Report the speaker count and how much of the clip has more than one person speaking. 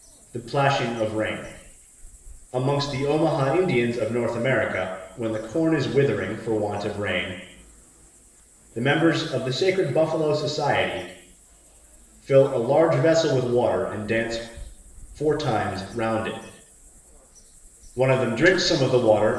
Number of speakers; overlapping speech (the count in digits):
1, no overlap